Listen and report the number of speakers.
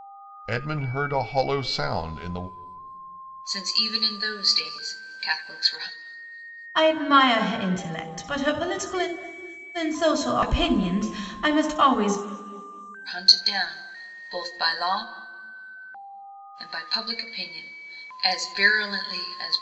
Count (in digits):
3